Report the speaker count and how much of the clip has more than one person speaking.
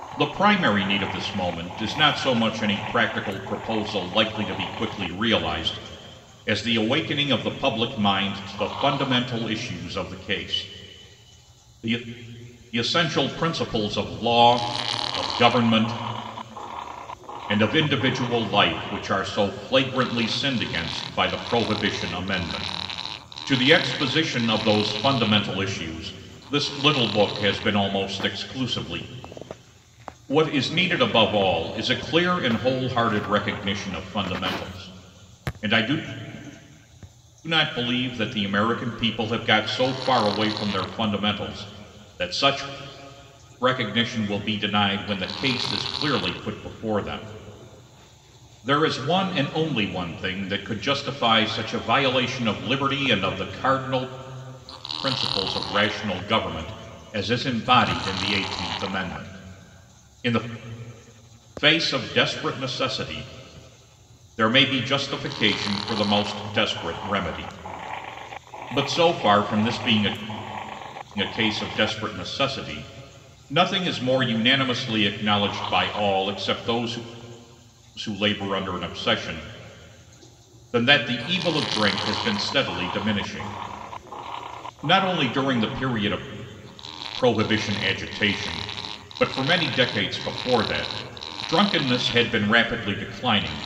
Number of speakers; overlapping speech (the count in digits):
1, no overlap